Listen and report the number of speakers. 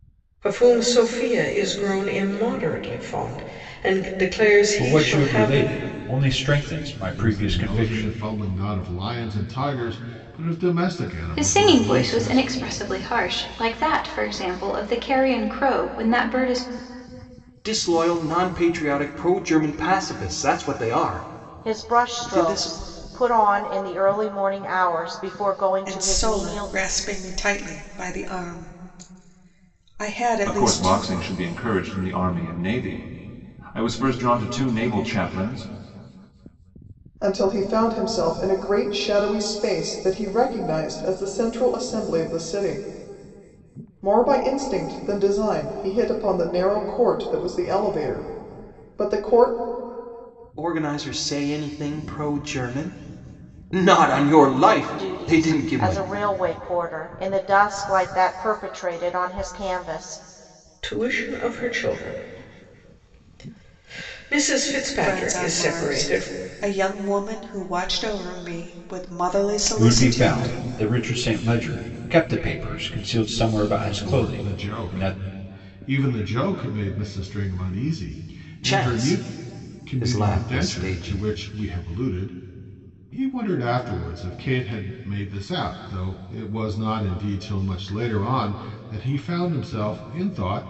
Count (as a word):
nine